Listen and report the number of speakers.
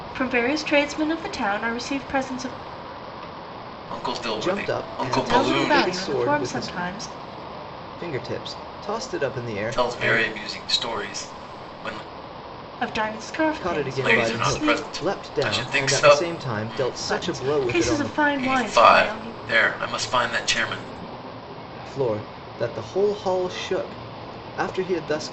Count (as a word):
three